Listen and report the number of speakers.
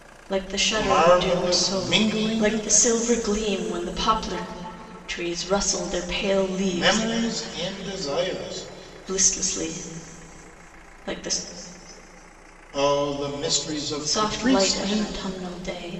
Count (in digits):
2